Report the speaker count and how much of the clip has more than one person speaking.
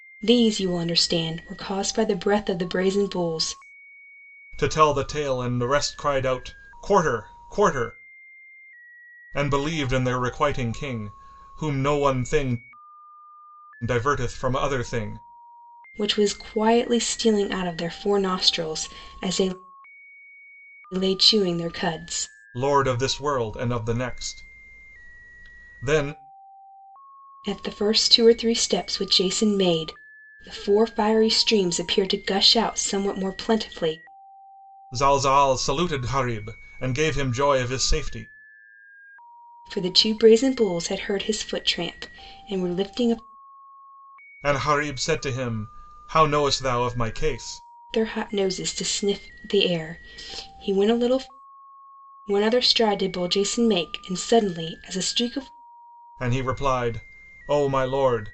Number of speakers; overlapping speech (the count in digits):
2, no overlap